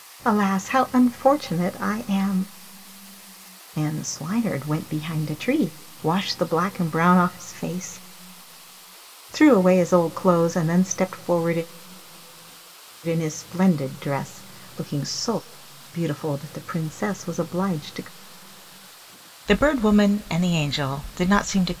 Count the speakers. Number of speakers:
one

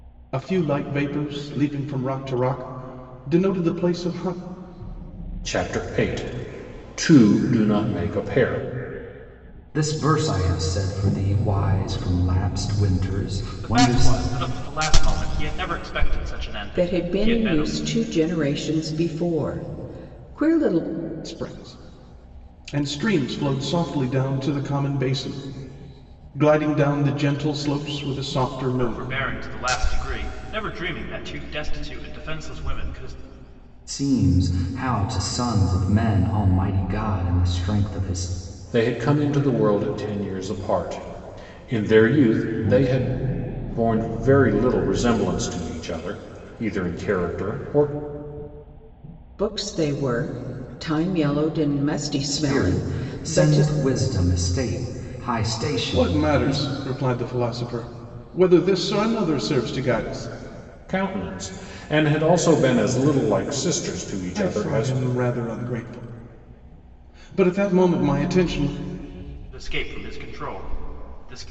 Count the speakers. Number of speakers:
five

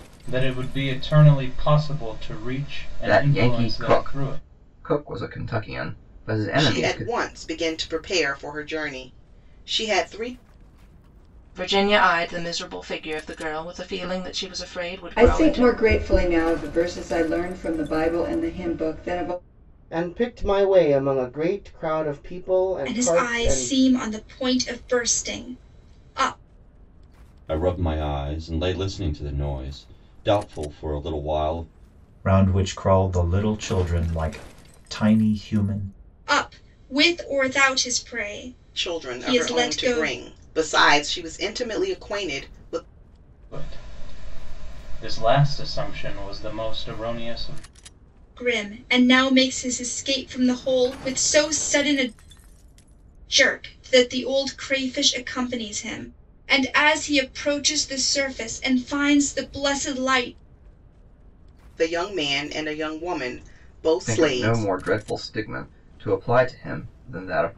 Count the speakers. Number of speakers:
nine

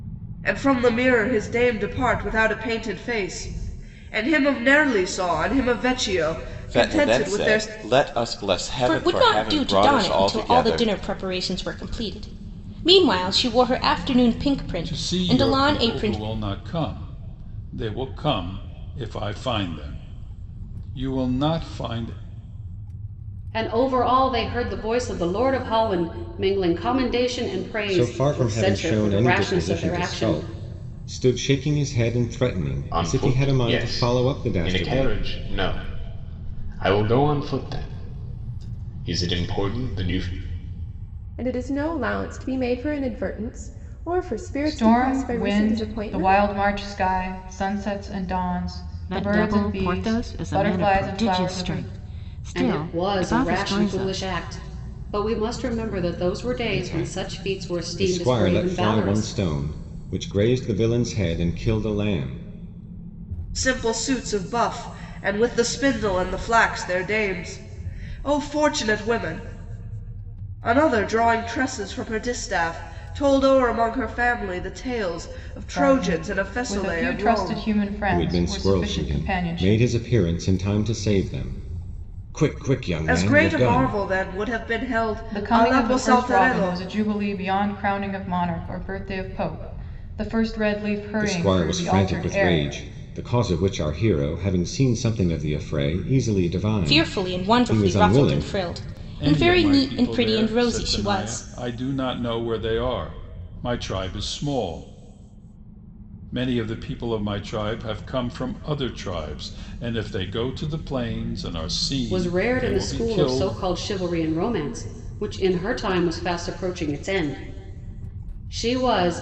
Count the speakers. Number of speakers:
ten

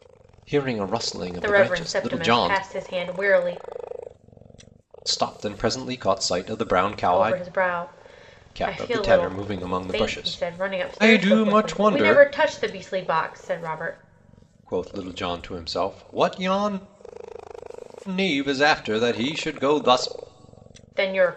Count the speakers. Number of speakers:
two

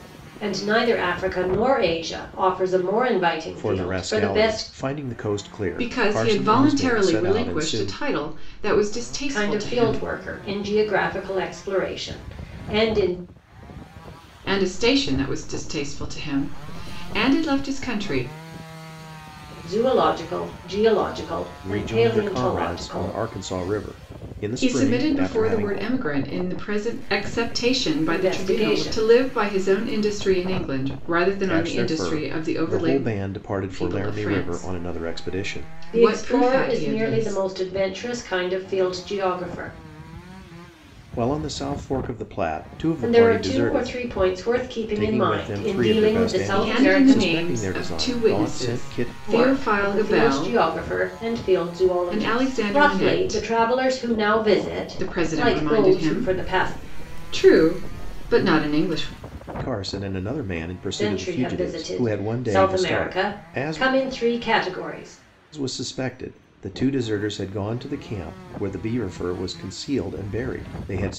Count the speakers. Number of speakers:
three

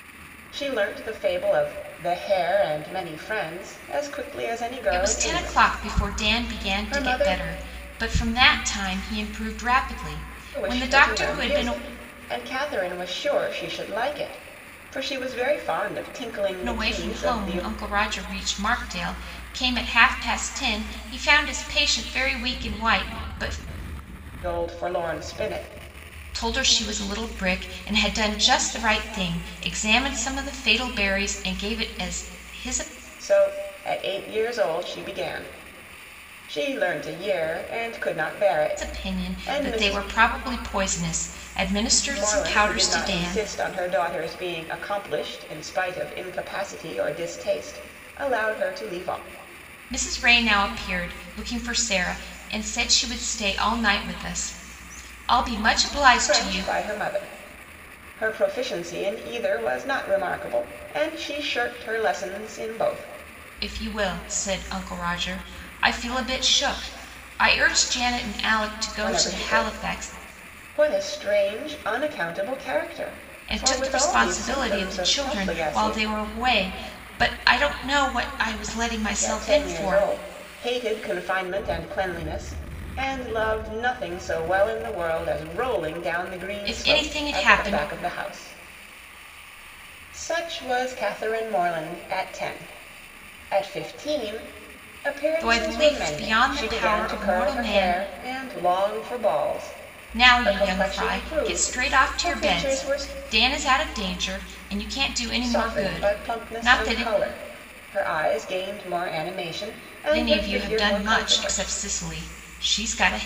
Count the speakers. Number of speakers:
two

